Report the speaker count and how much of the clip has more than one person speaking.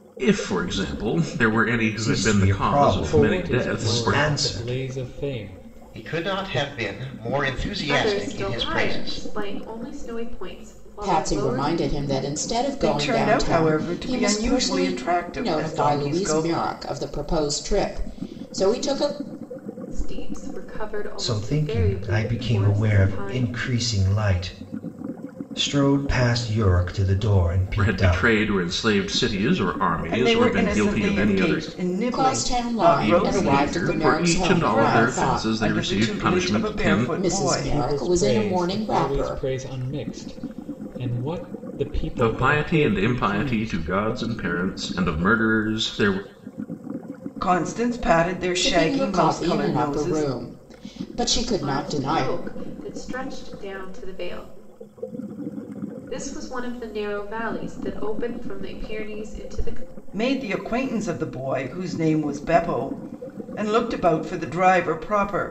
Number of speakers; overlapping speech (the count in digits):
7, about 39%